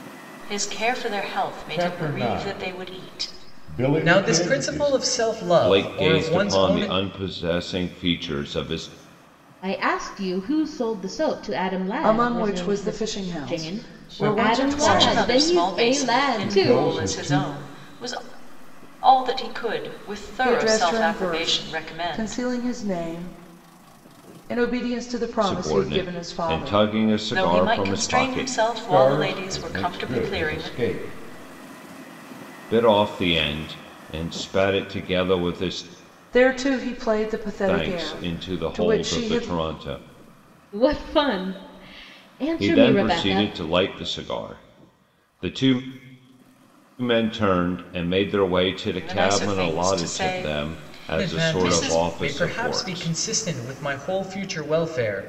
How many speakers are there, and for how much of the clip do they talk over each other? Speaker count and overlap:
six, about 41%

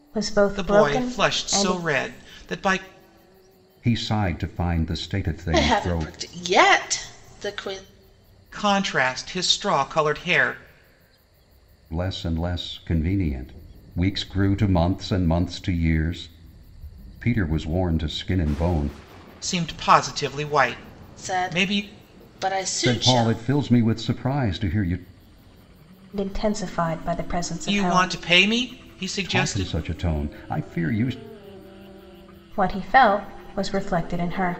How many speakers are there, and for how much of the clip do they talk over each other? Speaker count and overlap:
four, about 12%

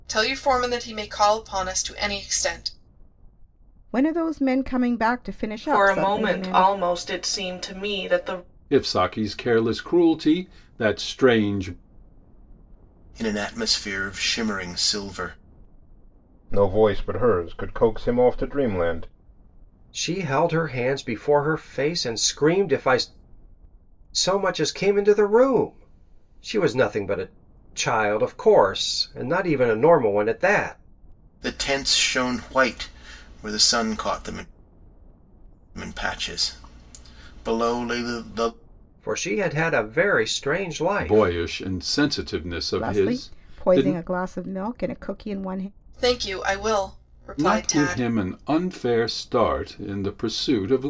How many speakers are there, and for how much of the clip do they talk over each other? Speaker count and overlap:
seven, about 7%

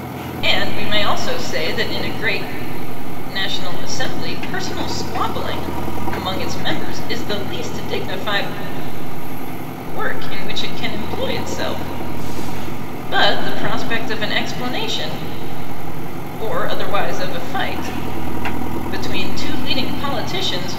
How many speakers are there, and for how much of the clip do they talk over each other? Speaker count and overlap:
one, no overlap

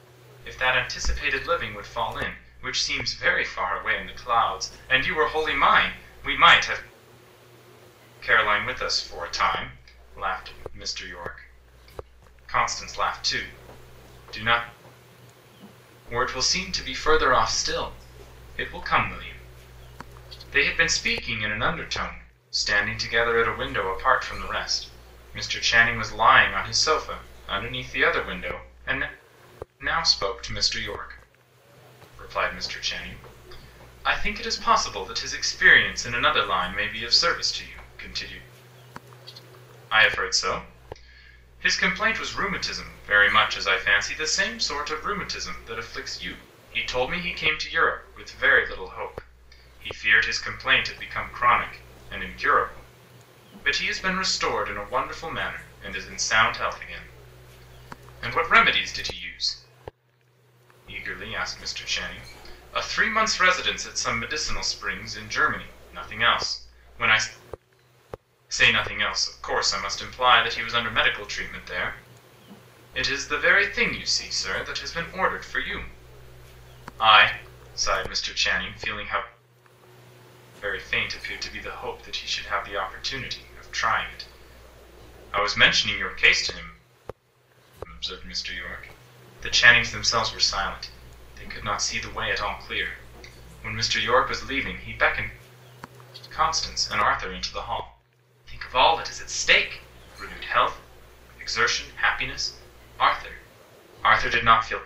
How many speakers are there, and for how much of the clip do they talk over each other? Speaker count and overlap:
one, no overlap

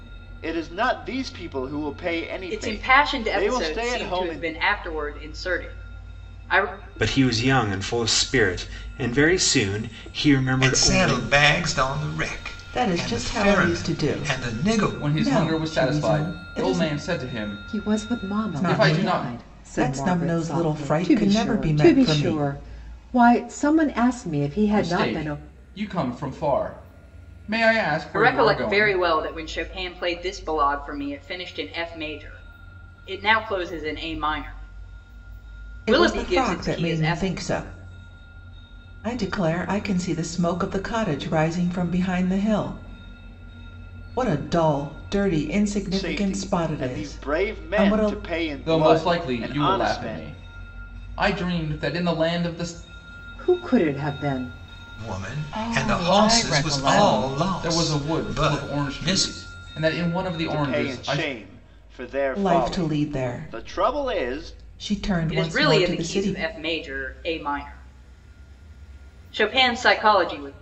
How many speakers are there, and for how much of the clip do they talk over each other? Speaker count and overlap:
seven, about 38%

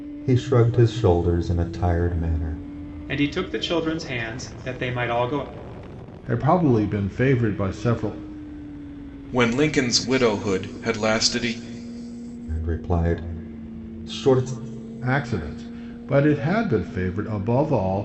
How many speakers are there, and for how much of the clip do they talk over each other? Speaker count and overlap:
four, no overlap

